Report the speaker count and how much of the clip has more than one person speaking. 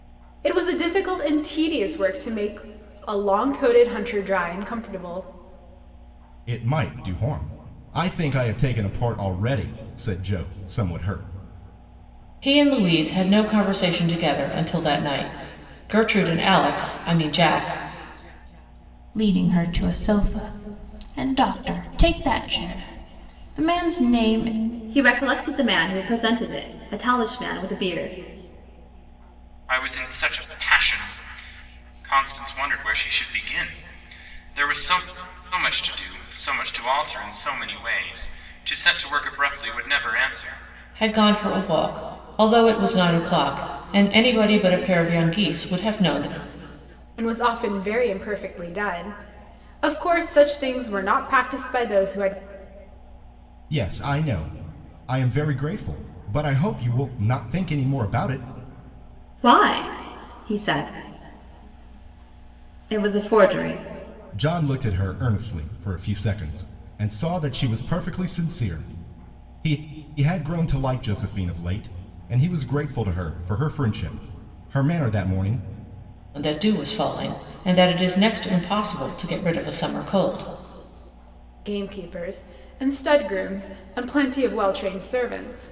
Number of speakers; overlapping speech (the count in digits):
6, no overlap